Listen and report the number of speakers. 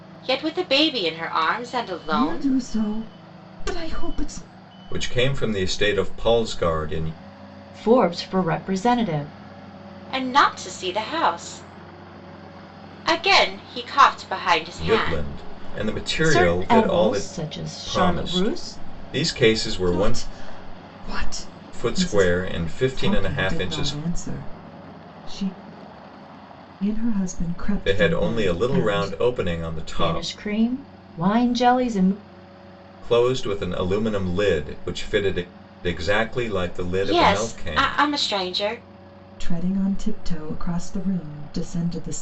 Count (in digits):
4